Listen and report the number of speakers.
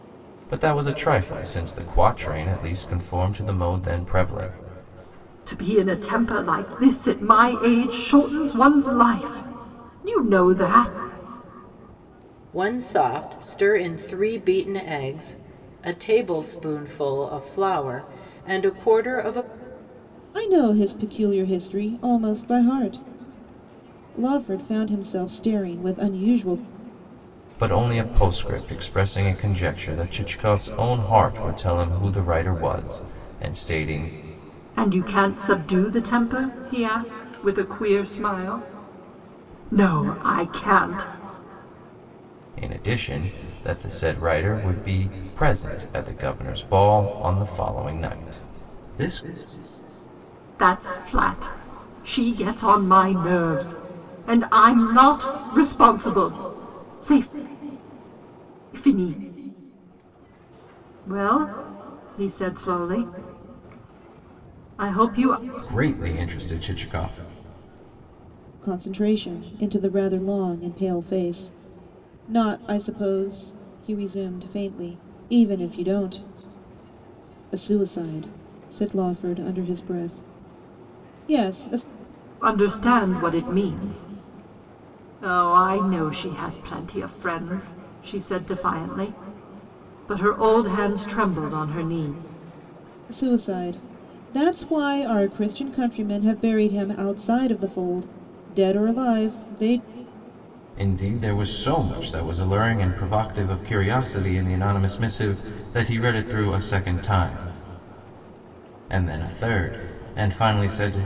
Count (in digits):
4